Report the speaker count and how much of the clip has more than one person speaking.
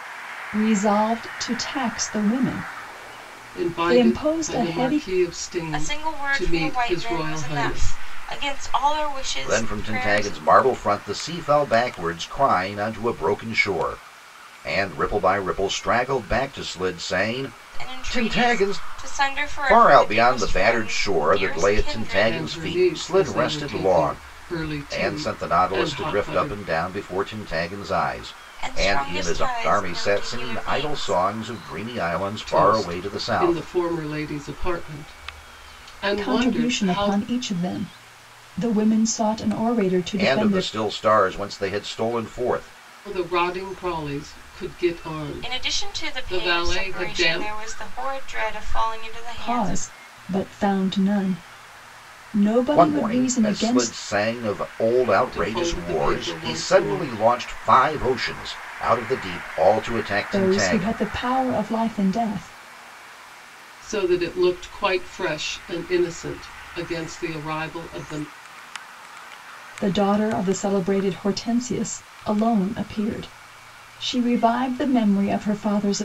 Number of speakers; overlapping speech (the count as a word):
four, about 32%